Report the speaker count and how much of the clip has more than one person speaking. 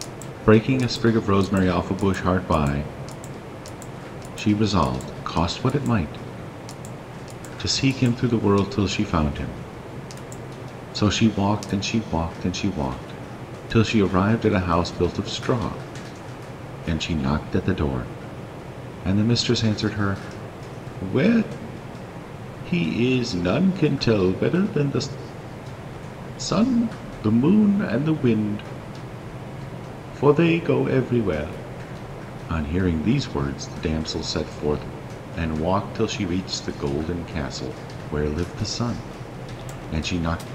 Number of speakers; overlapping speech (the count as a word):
one, no overlap